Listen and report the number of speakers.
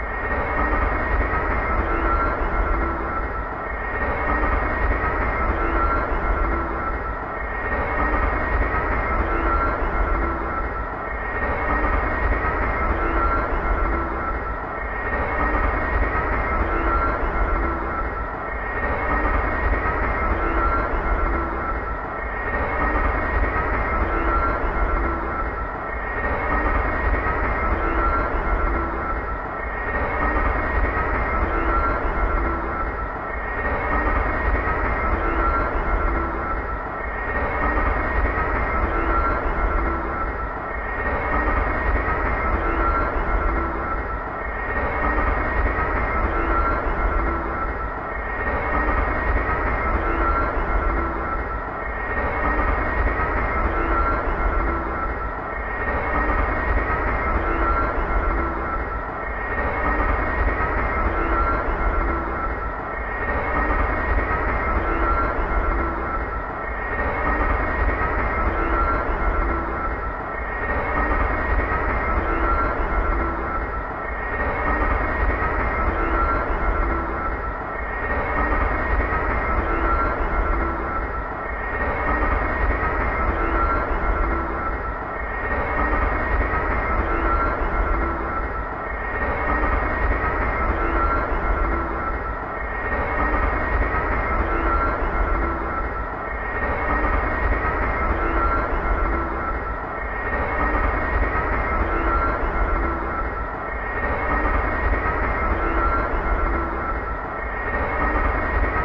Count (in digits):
0